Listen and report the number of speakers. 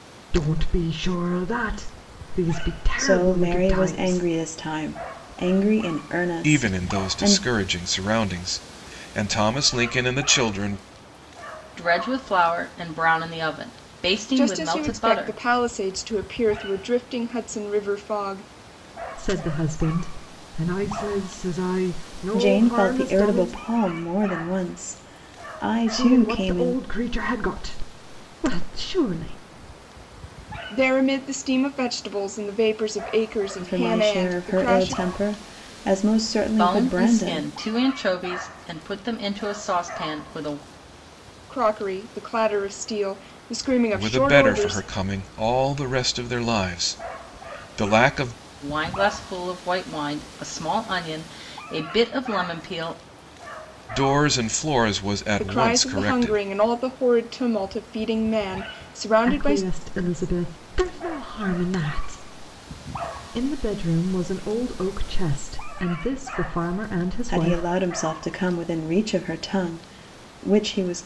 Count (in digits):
5